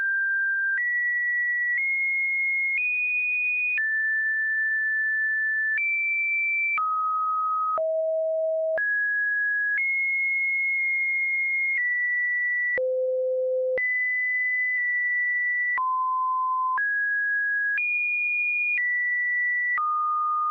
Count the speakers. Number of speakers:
0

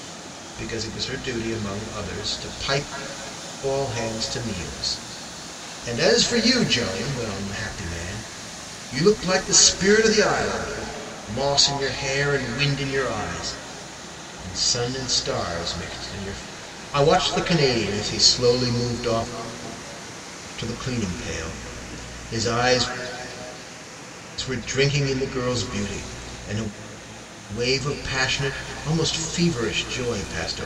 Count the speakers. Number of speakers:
1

